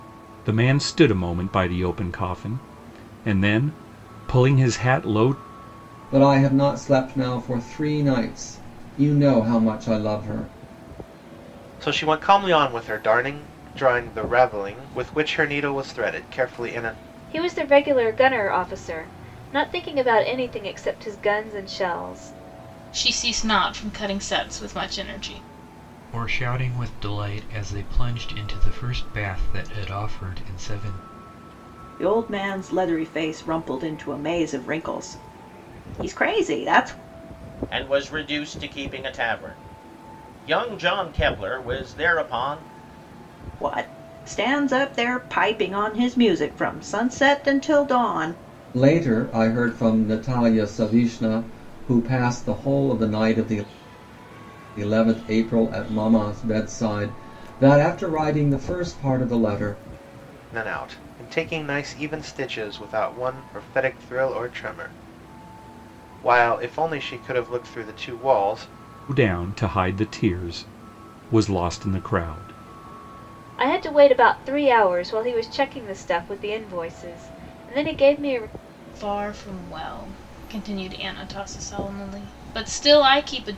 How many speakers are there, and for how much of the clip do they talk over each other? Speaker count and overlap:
8, no overlap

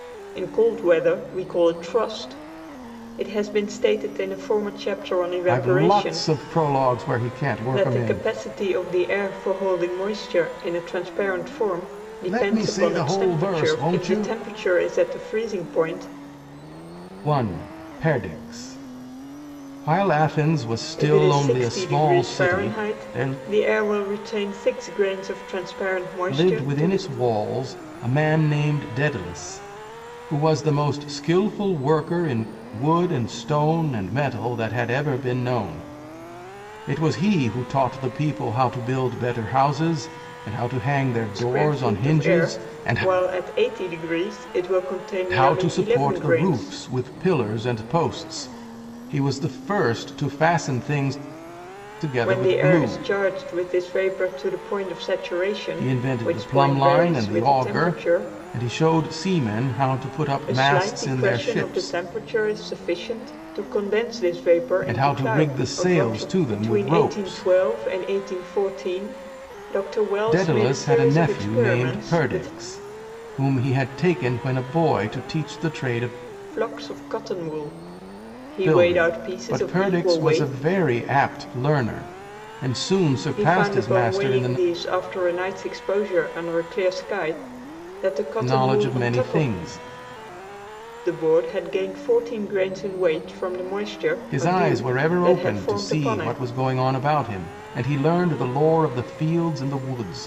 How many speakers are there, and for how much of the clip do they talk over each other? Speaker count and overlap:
2, about 26%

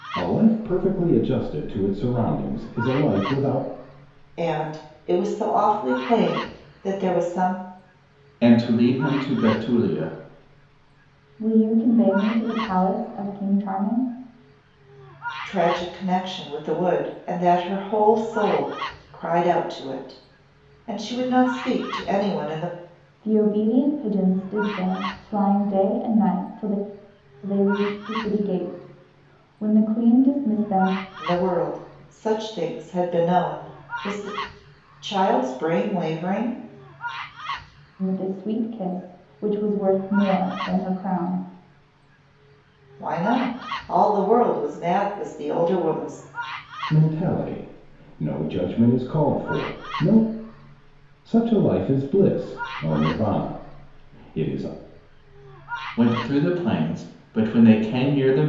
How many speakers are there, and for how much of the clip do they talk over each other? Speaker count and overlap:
4, no overlap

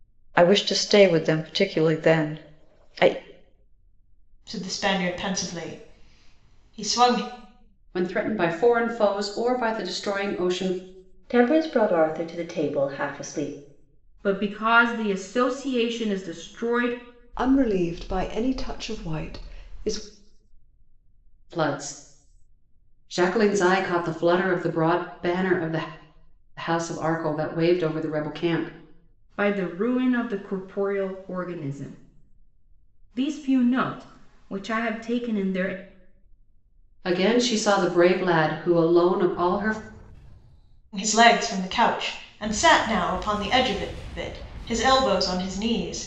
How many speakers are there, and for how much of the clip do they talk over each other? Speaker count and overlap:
6, no overlap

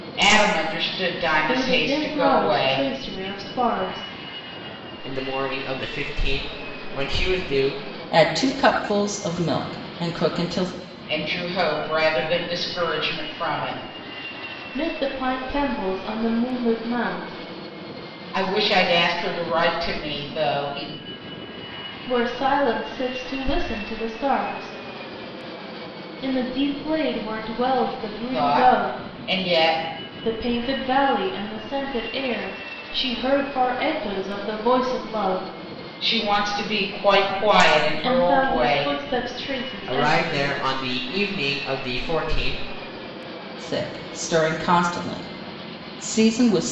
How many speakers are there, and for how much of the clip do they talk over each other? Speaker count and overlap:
4, about 9%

